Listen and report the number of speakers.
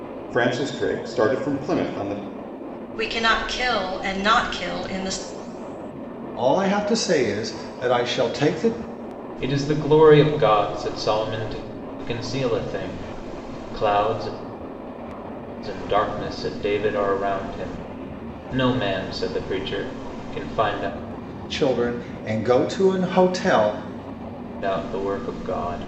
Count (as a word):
four